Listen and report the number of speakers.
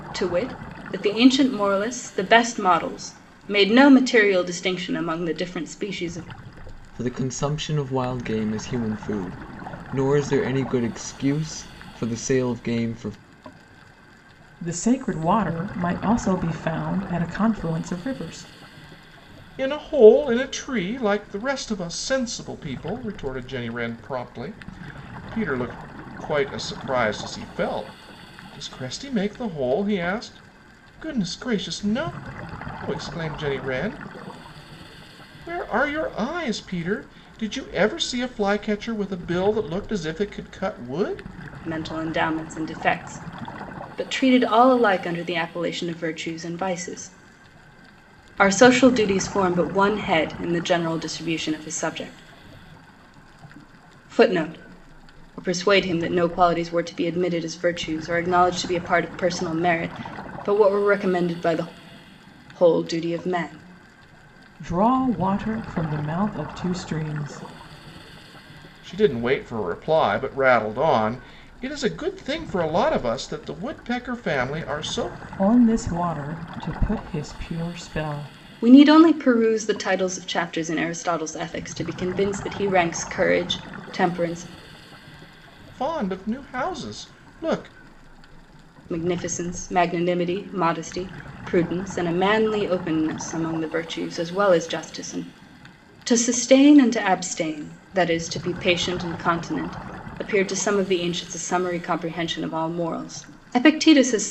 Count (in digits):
4